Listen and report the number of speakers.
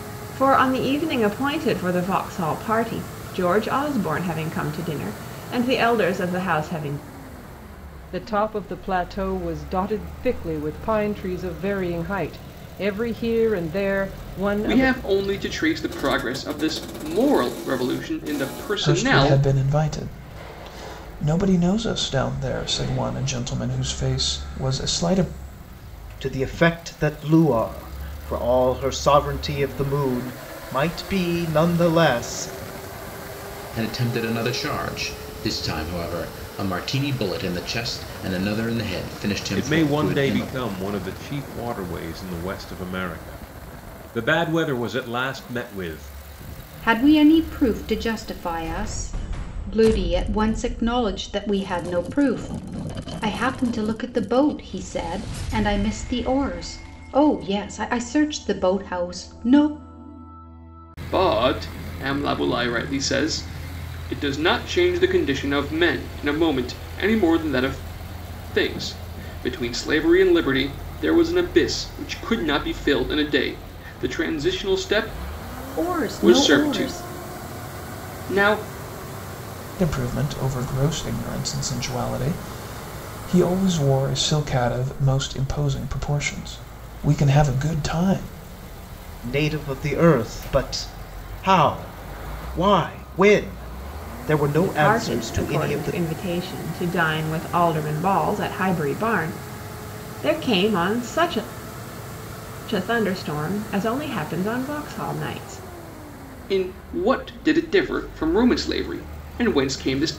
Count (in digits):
8